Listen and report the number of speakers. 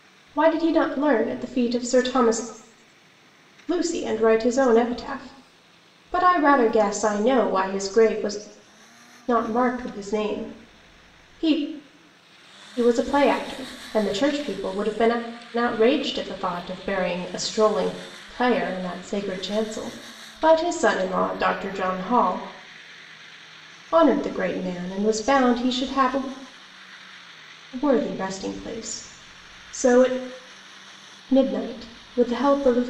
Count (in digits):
1